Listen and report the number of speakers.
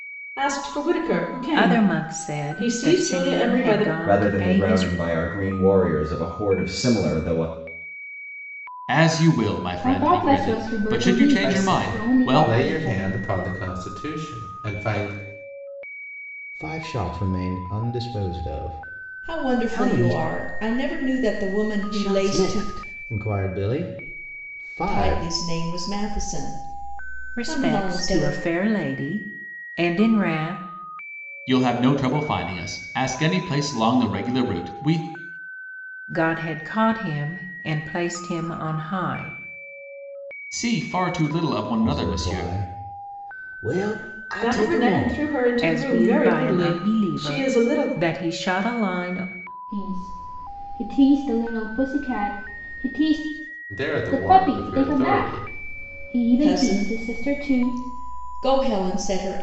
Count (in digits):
8